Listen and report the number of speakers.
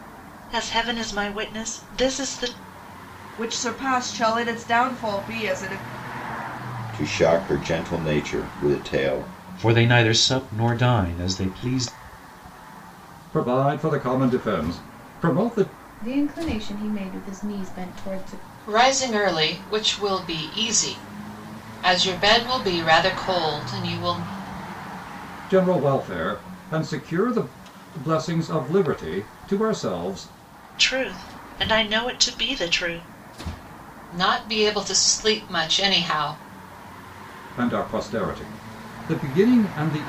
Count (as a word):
seven